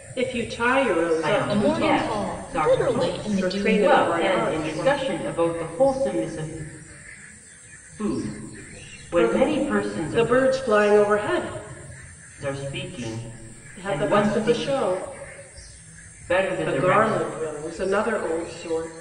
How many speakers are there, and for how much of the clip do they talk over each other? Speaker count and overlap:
three, about 34%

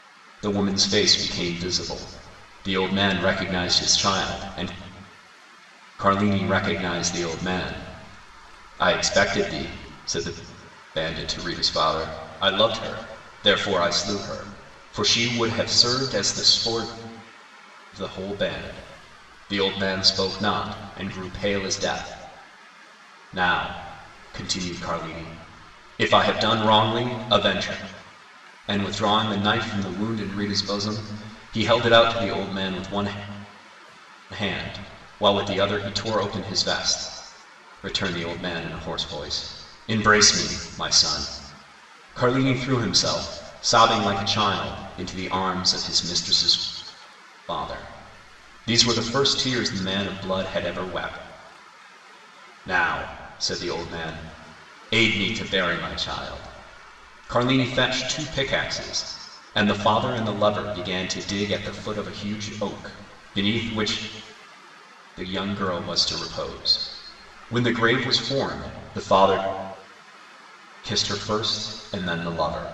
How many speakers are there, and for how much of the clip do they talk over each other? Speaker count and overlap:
one, no overlap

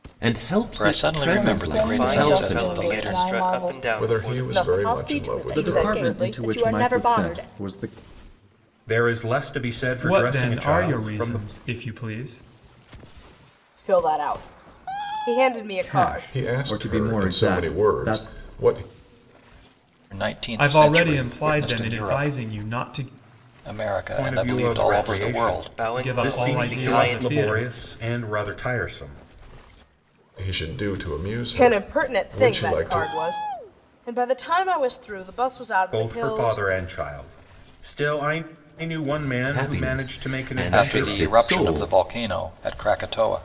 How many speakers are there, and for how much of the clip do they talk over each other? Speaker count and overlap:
ten, about 48%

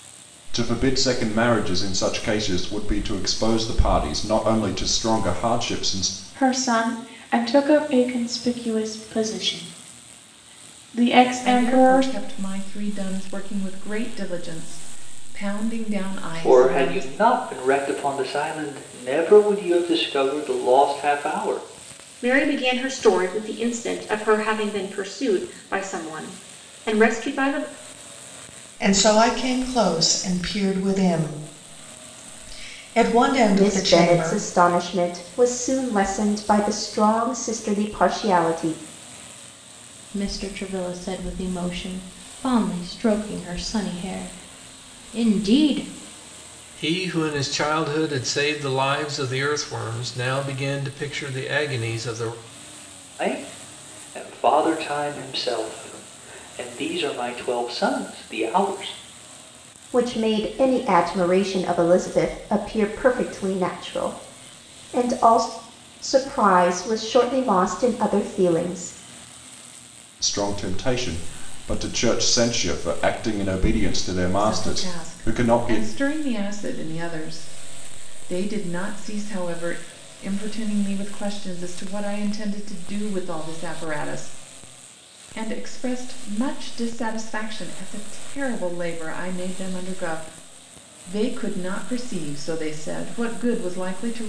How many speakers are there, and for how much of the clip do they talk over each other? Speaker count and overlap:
nine, about 4%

